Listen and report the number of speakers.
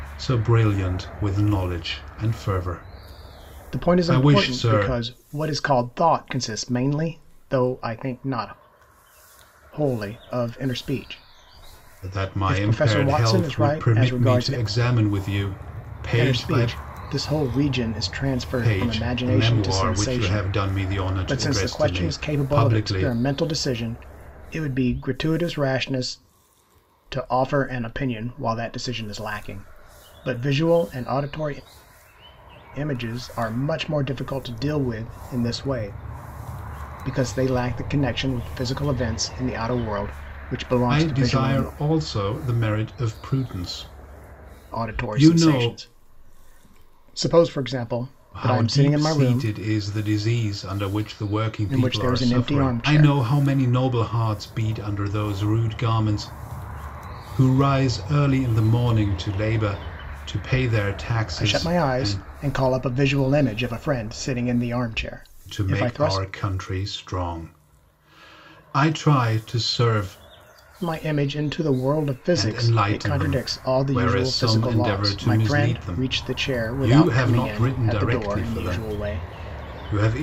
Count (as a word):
two